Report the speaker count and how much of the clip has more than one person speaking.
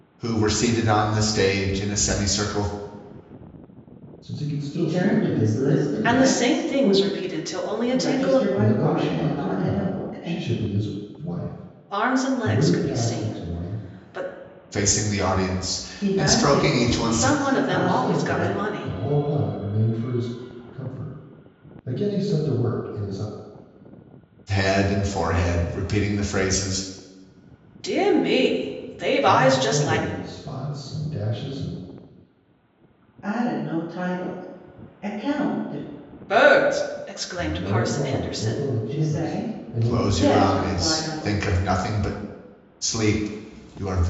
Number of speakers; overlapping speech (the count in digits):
4, about 33%